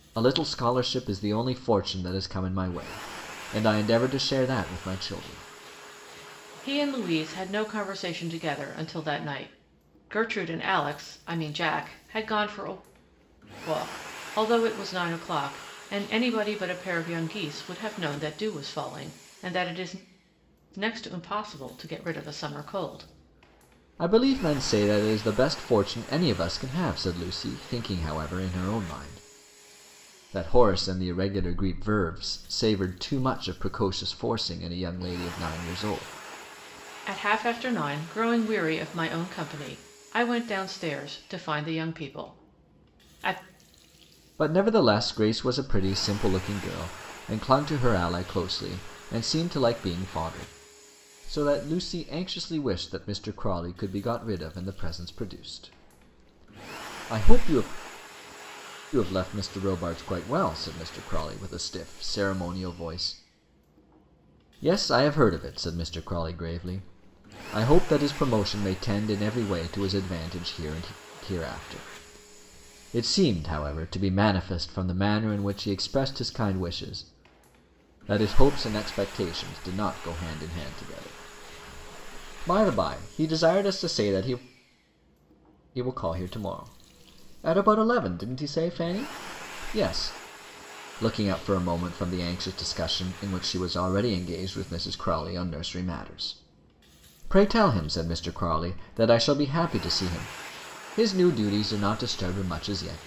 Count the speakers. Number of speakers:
two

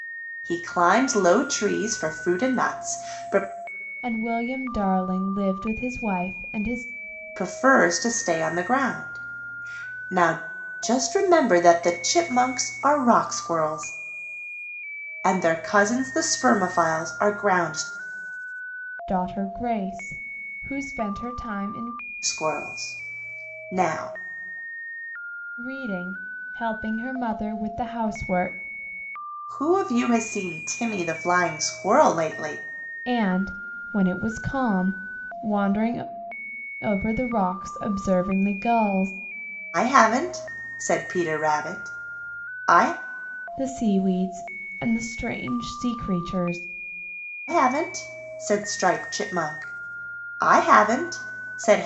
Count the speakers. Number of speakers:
two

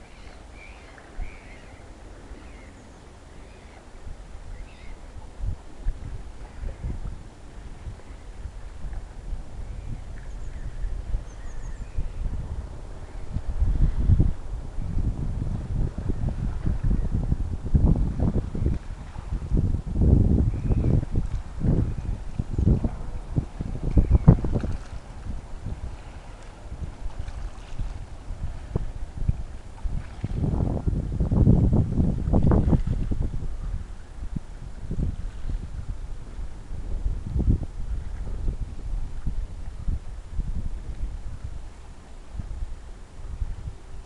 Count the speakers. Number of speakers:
zero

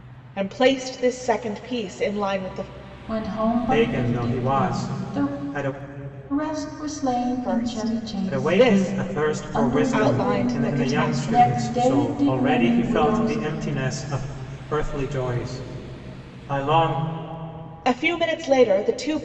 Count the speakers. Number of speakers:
three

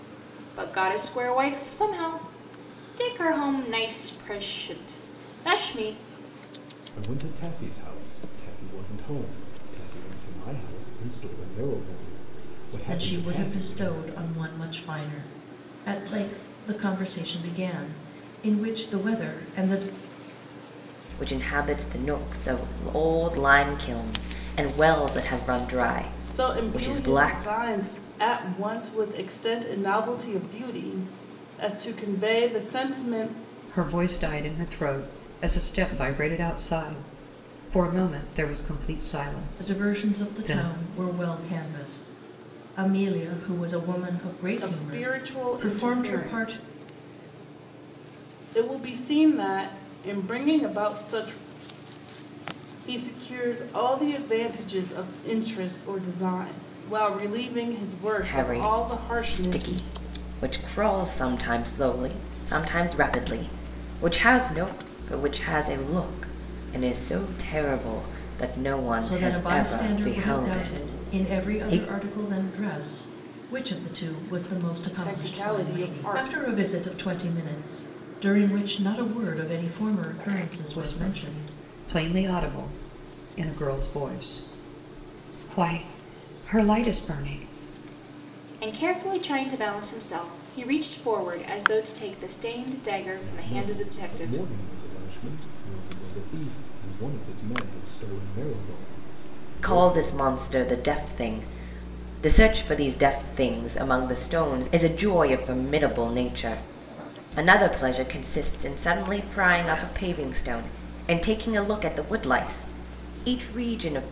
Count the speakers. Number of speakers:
six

